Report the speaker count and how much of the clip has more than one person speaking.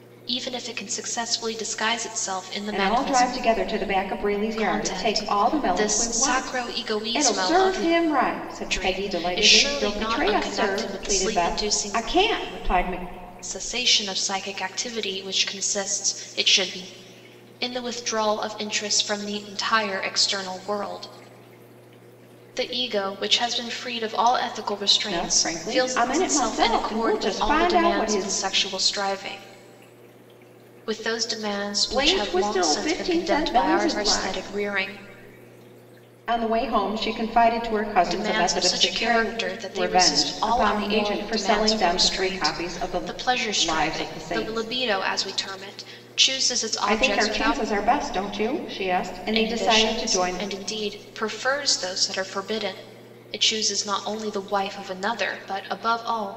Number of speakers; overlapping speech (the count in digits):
2, about 37%